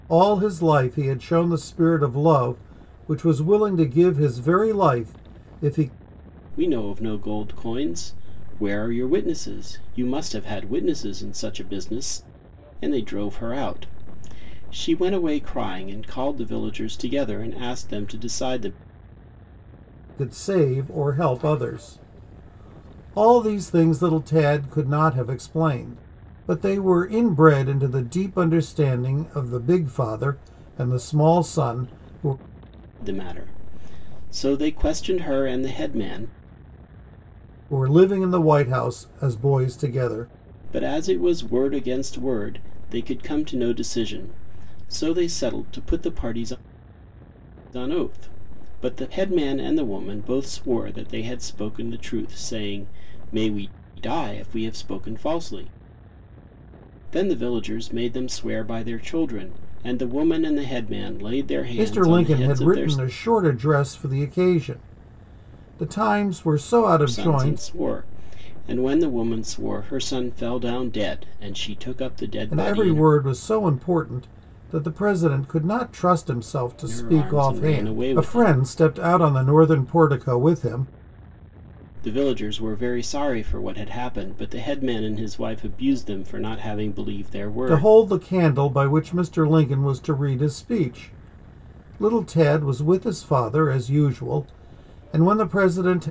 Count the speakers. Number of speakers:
2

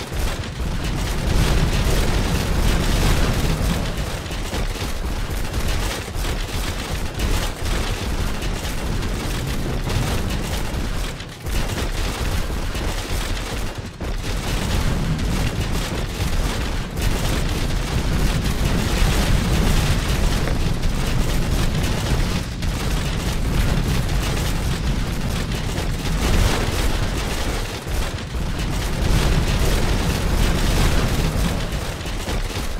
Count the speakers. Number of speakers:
0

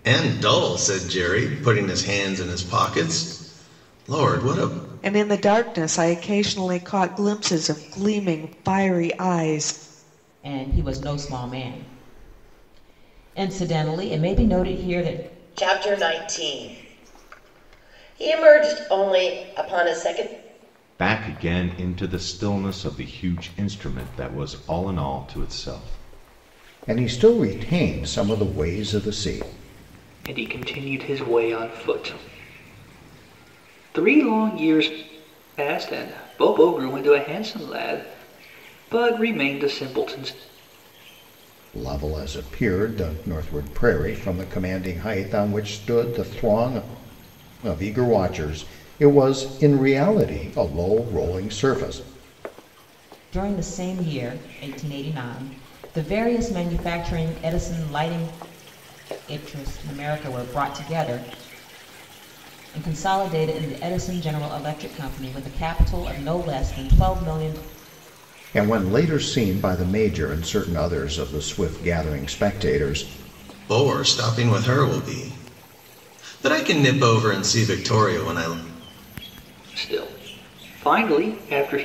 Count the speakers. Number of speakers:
7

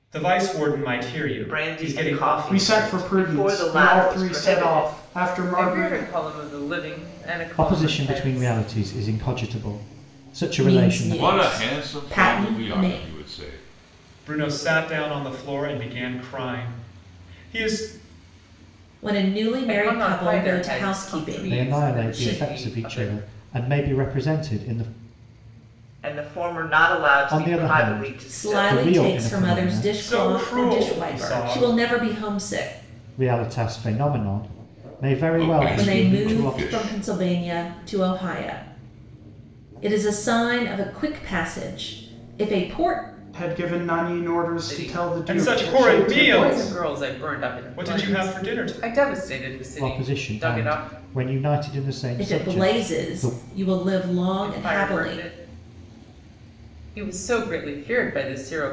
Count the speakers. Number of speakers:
7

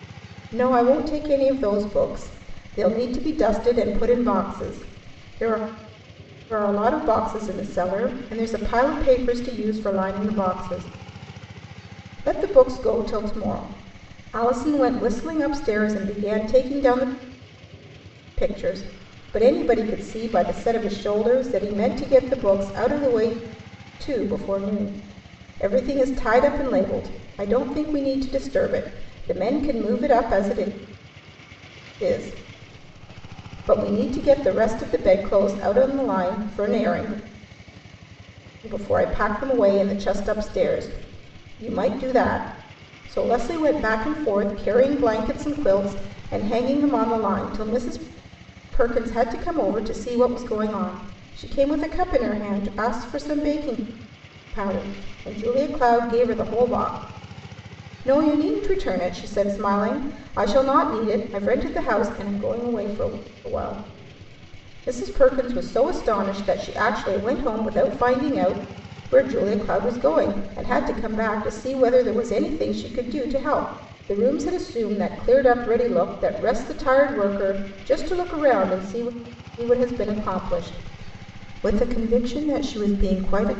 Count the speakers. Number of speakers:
1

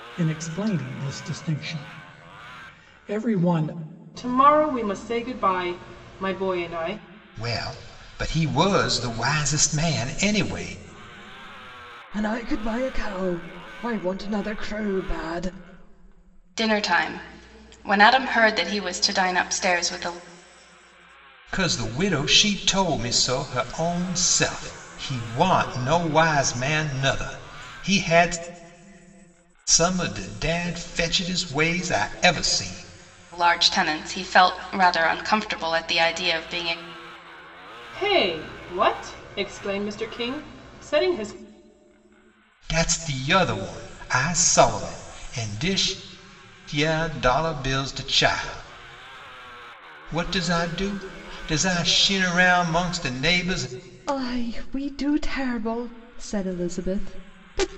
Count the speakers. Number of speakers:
5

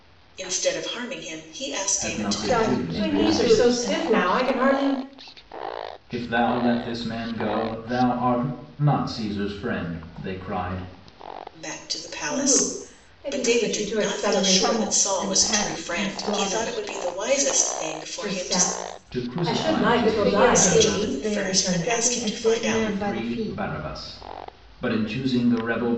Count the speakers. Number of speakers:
4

